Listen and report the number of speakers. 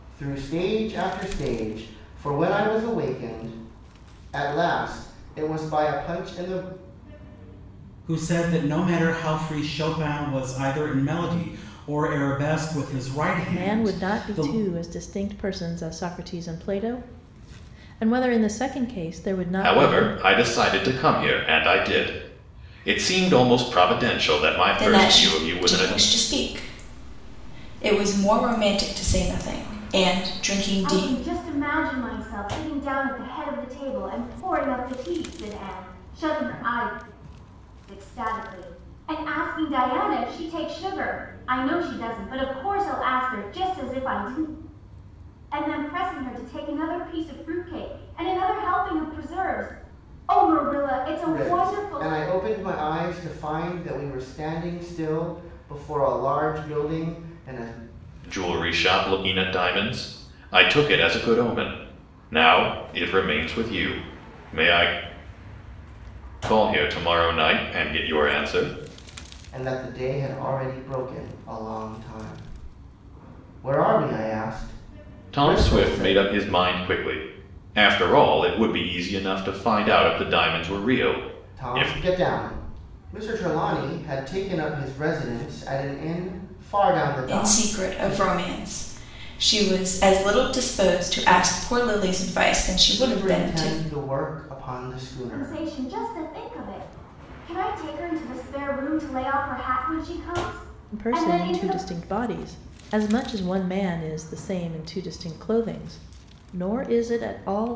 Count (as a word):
six